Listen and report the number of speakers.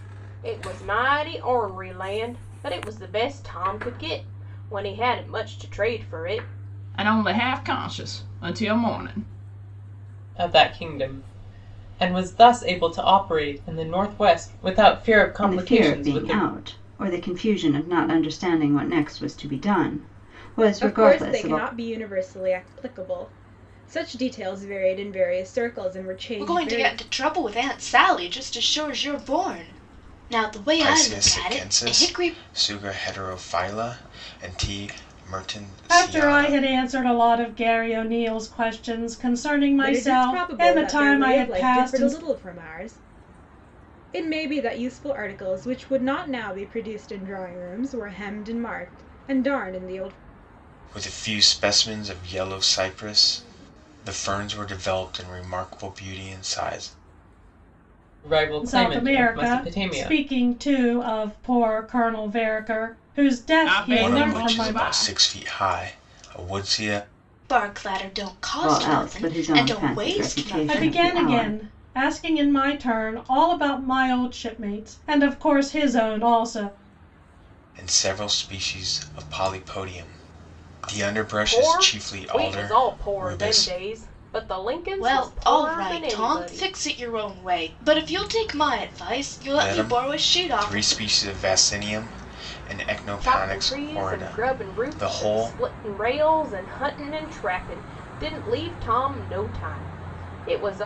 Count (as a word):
eight